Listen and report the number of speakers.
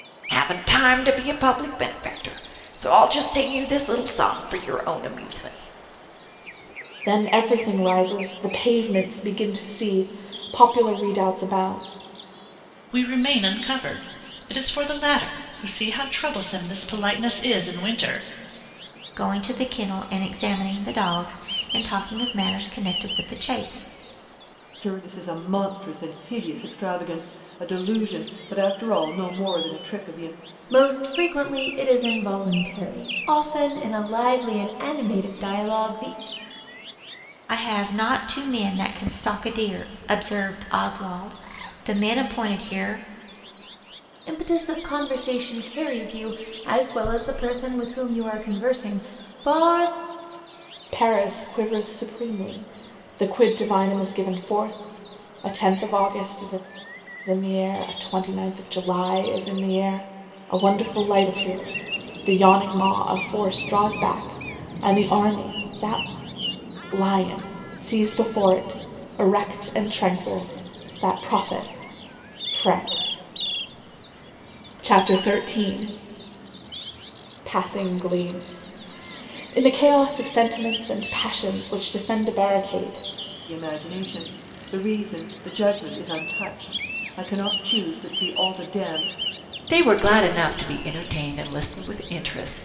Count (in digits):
6